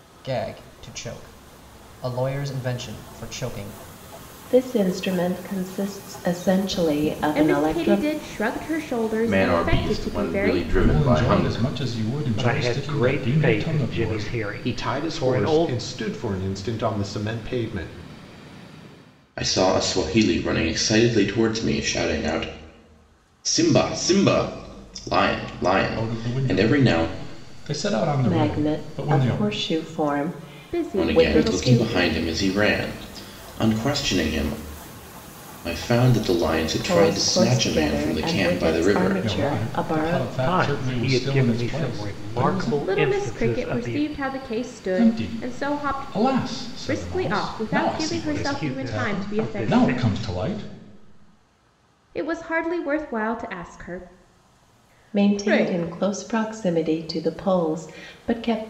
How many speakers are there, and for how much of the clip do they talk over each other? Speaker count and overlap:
7, about 39%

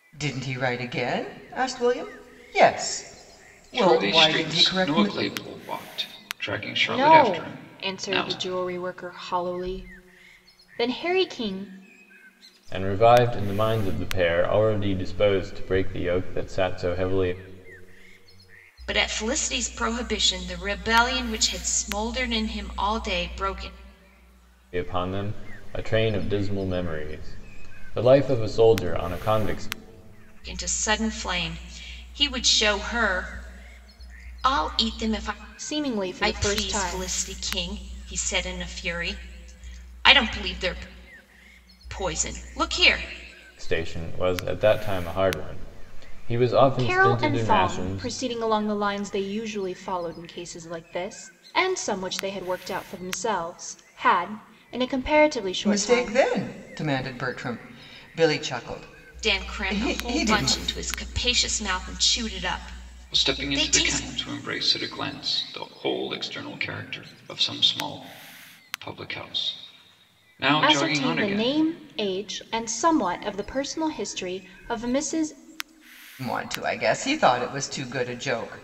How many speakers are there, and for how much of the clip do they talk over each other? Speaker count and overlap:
5, about 12%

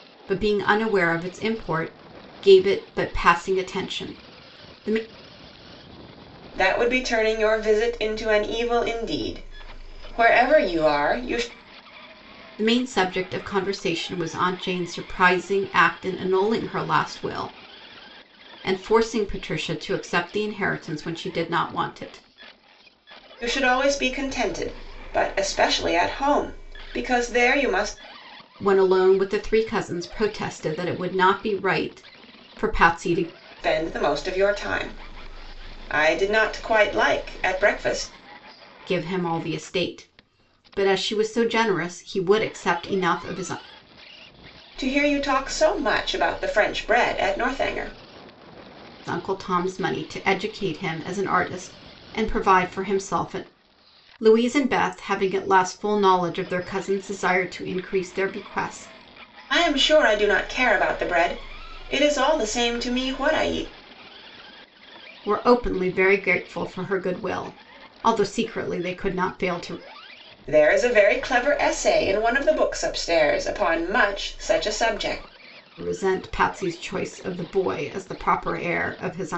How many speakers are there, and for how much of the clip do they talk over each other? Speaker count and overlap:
2, no overlap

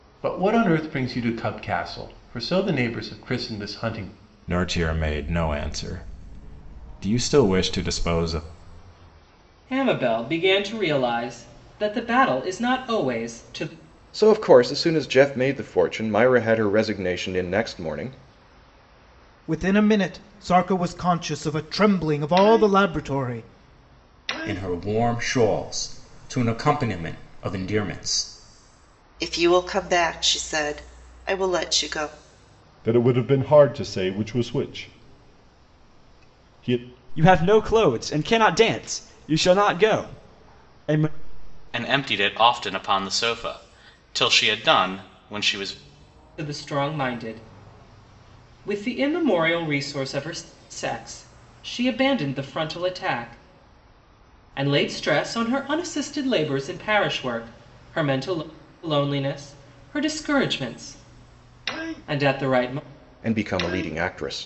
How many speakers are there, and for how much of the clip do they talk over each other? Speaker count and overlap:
10, no overlap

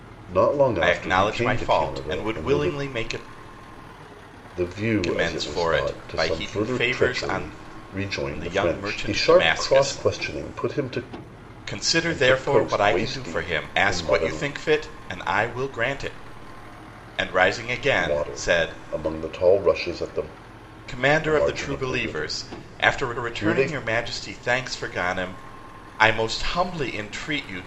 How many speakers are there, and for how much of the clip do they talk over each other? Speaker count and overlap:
2, about 43%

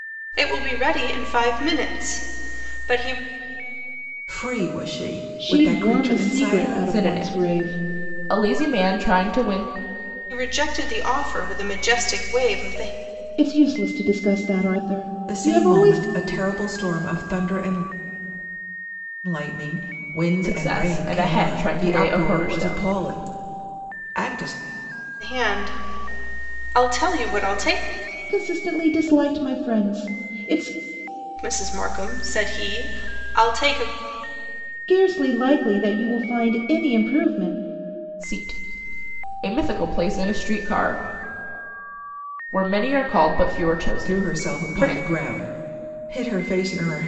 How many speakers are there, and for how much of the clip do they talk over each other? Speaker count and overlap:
4, about 15%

